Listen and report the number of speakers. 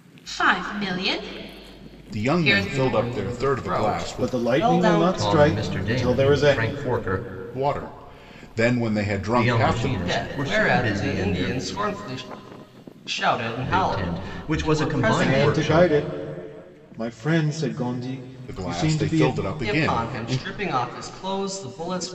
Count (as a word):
five